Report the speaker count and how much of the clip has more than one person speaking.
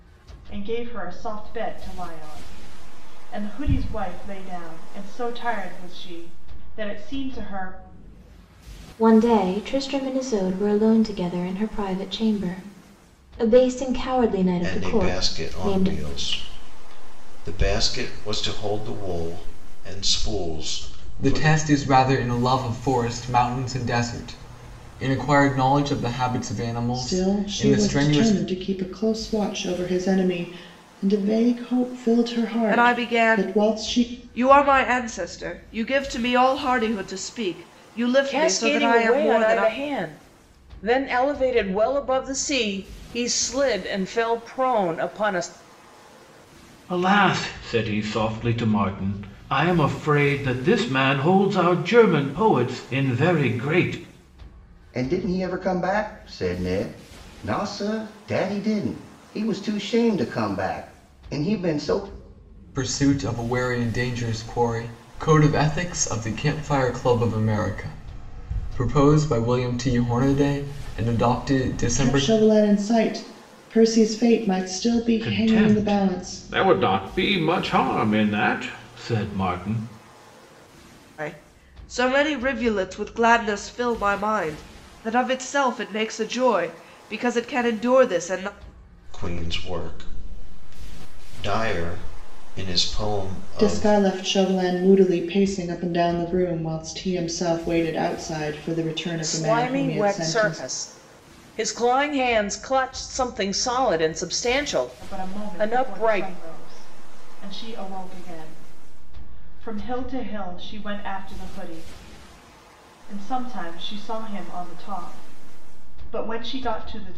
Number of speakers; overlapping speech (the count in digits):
9, about 10%